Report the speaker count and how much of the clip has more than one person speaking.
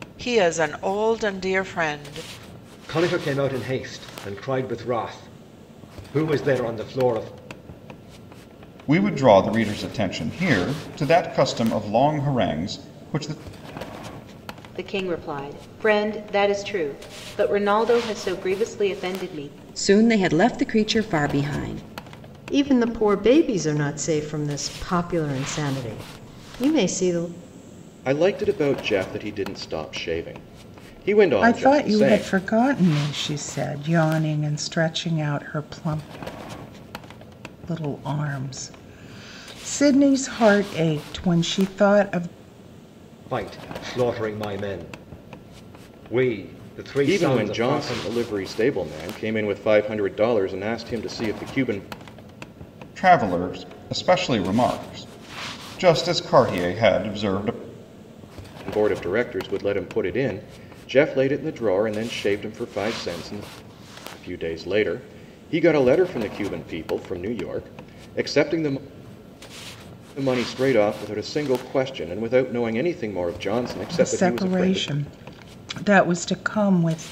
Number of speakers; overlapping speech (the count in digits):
8, about 4%